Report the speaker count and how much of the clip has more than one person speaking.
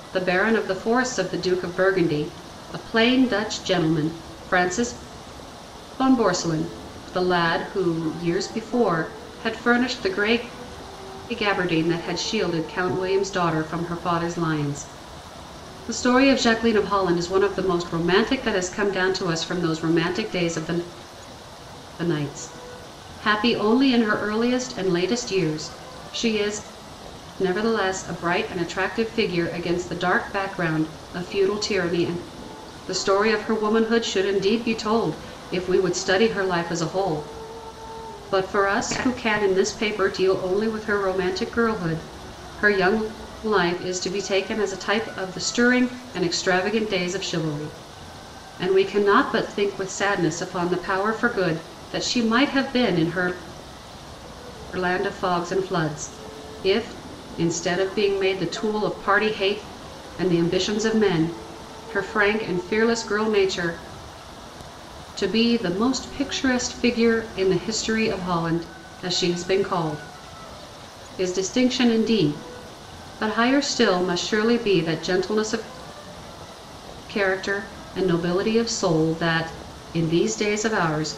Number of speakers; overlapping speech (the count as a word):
one, no overlap